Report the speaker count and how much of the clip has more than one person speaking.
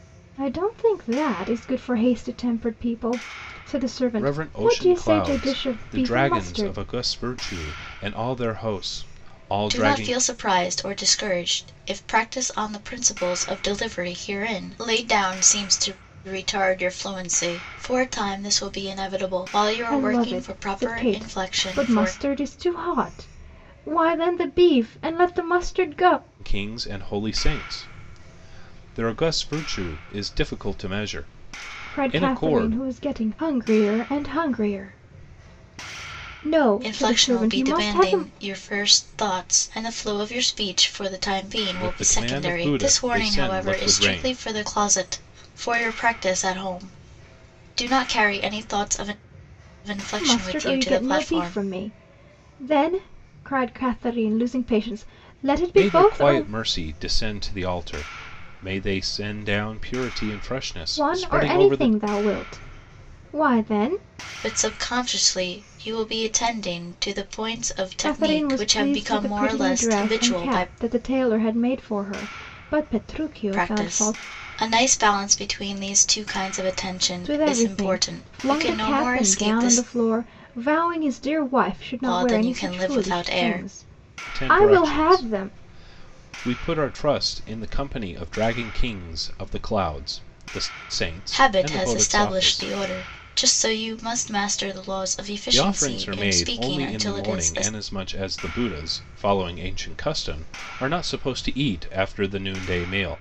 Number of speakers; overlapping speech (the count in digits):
3, about 26%